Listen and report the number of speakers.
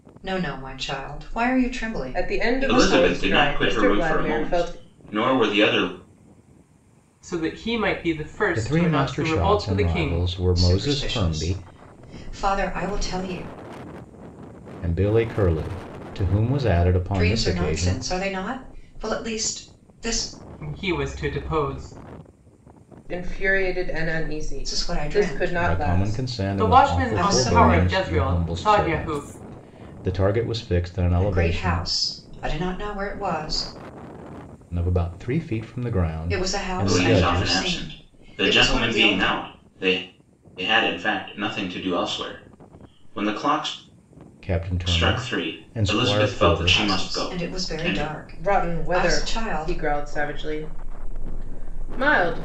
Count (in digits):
5